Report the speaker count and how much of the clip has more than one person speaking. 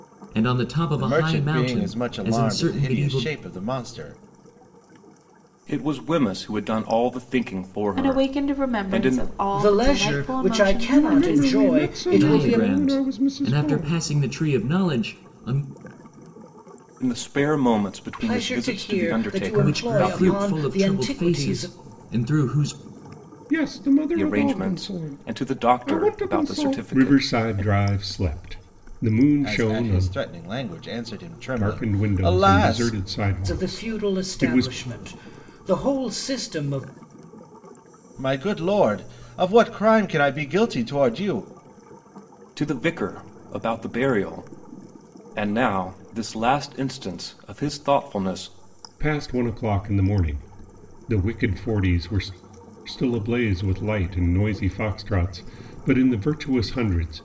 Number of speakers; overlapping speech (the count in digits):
6, about 33%